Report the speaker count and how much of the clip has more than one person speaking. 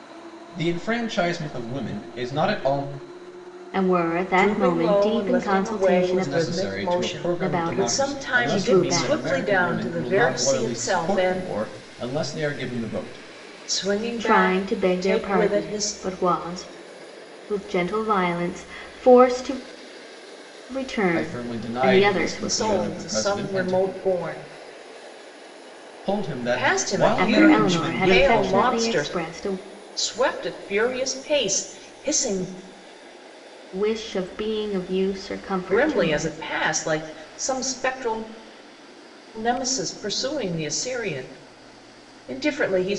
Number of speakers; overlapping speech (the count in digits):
3, about 35%